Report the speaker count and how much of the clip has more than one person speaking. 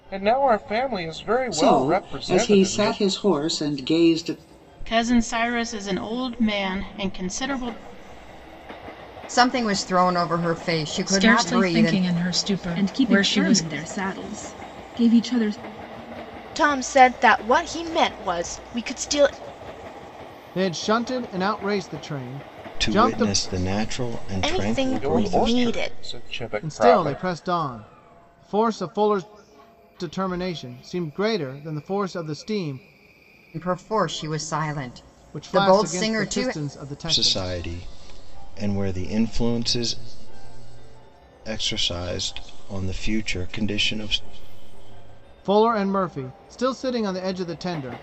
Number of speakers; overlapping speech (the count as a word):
nine, about 17%